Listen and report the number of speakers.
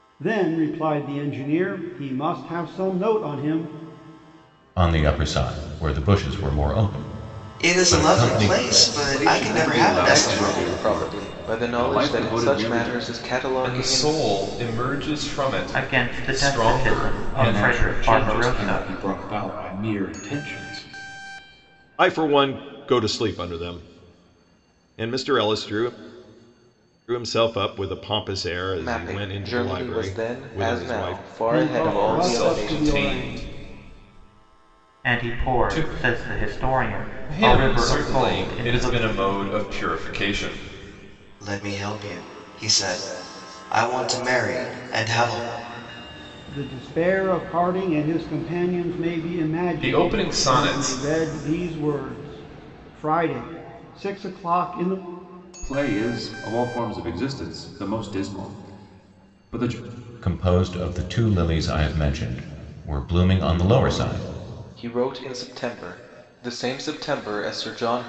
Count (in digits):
9